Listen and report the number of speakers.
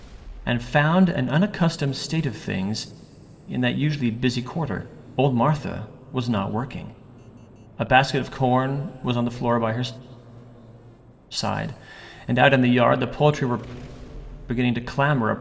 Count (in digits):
1